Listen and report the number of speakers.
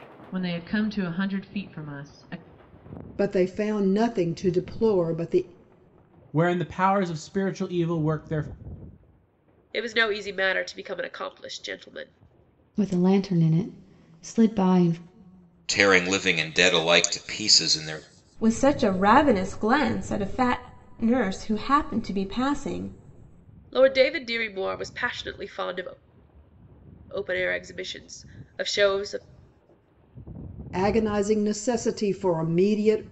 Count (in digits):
7